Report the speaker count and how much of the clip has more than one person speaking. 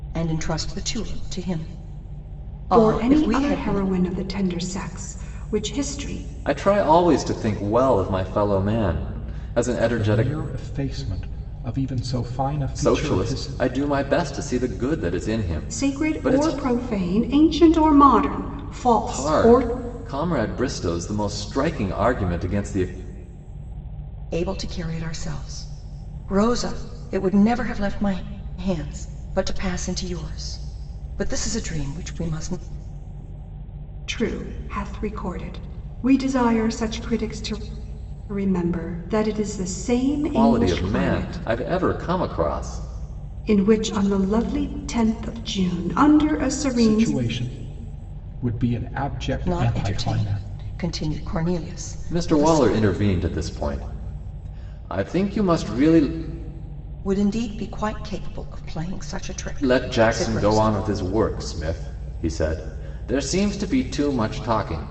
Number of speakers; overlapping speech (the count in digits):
4, about 13%